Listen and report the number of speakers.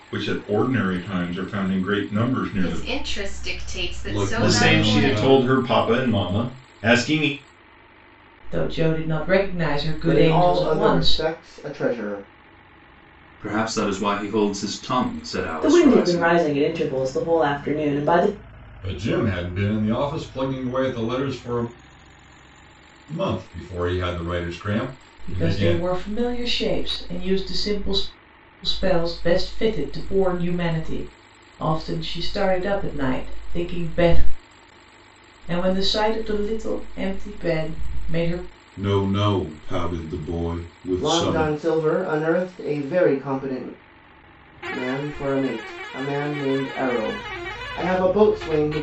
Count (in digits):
9